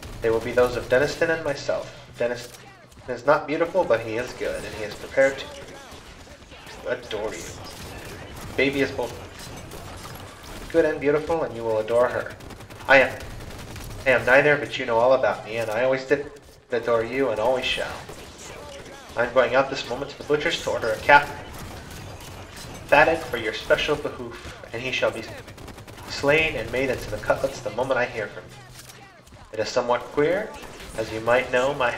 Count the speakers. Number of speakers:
1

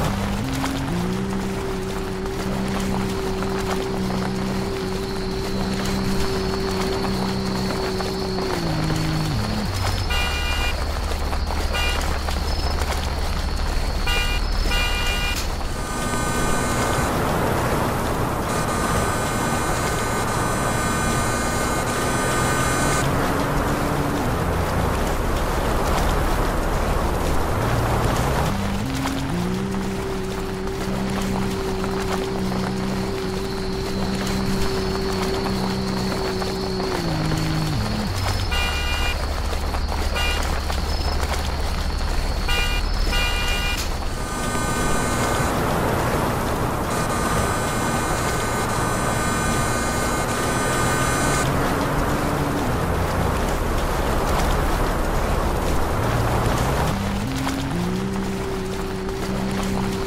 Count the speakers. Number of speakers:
0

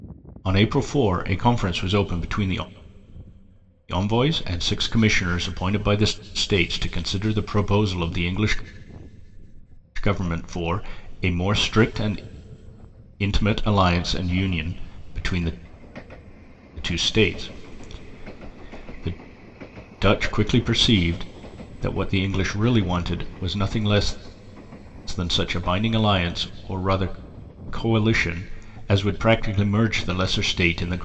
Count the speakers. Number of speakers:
1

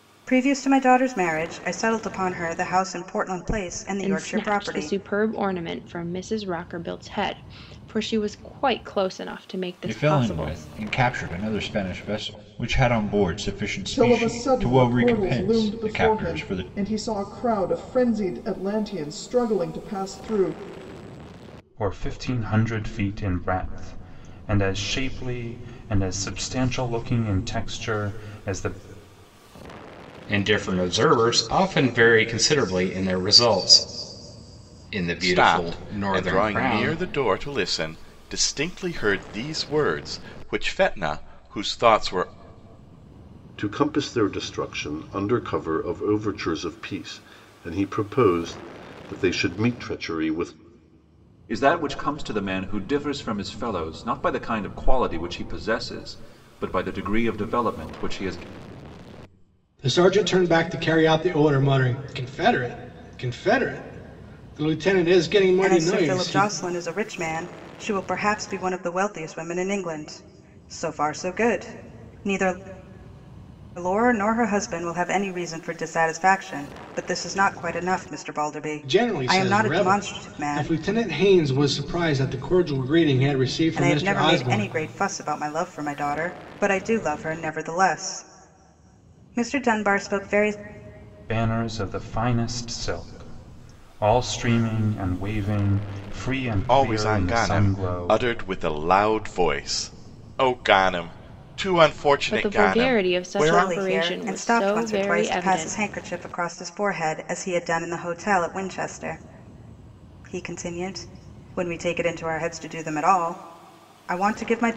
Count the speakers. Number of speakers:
10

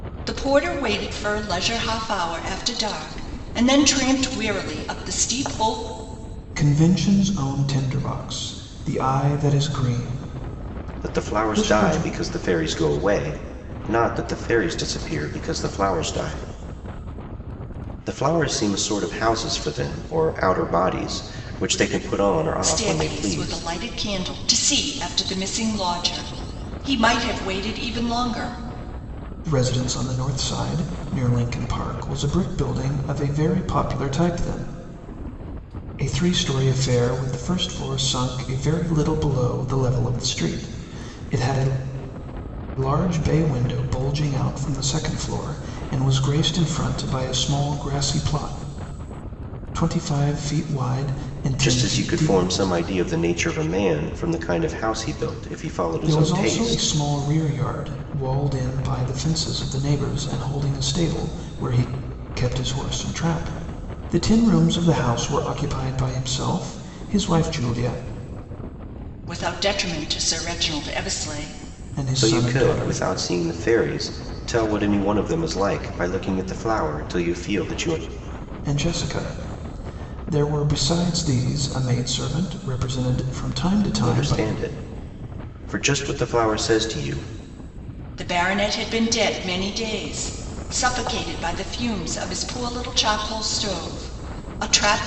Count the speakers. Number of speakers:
3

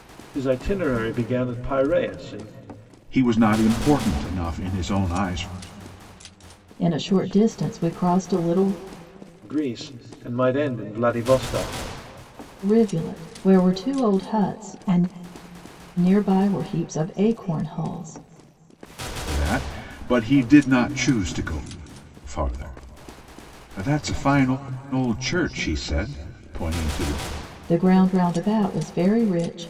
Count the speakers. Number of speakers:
3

